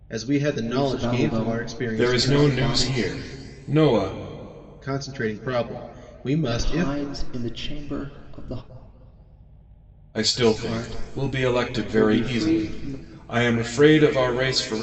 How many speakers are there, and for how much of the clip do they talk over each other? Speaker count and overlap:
three, about 36%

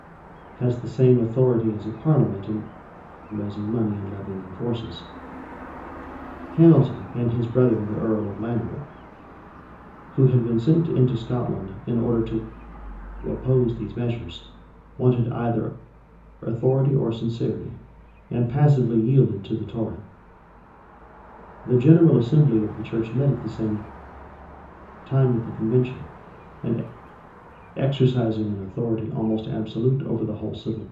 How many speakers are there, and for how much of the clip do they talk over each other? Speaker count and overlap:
one, no overlap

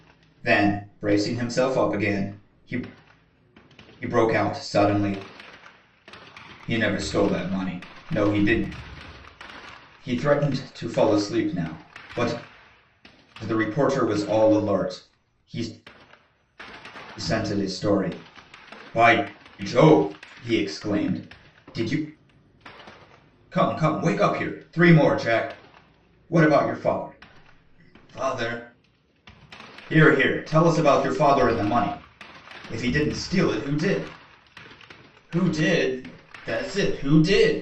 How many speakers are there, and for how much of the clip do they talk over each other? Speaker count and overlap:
one, no overlap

